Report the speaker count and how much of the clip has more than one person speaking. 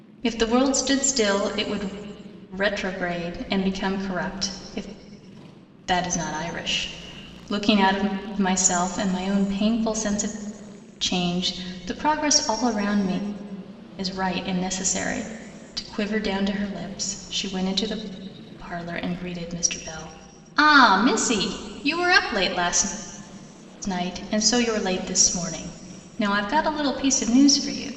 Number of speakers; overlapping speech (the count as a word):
one, no overlap